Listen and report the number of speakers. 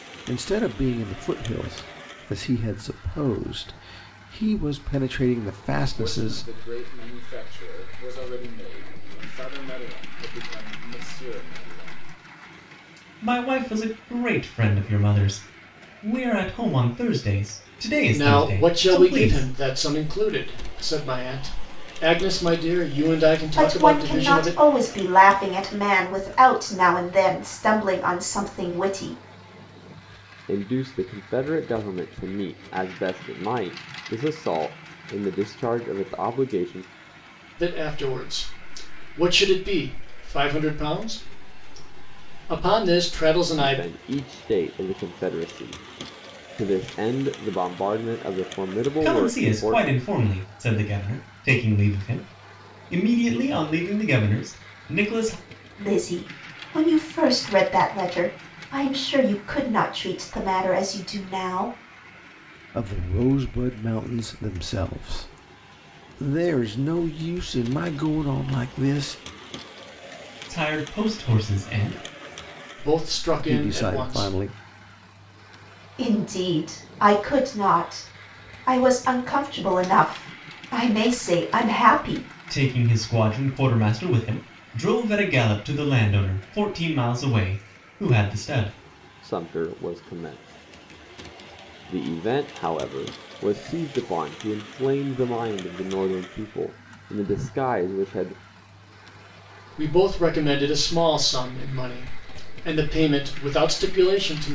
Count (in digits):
6